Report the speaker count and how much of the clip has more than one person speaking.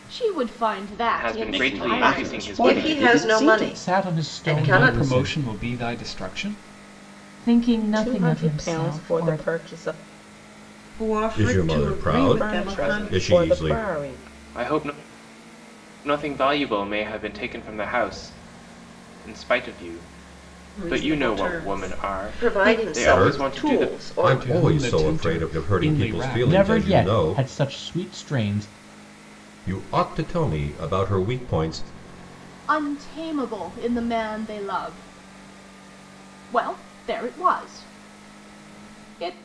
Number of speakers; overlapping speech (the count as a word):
ten, about 39%